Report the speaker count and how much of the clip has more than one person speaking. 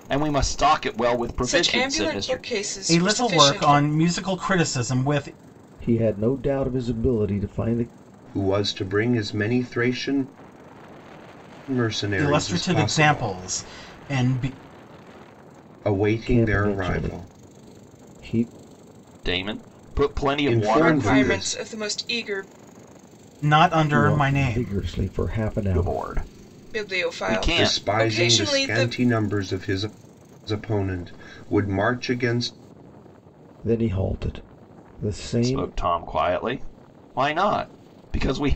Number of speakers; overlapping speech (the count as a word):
five, about 24%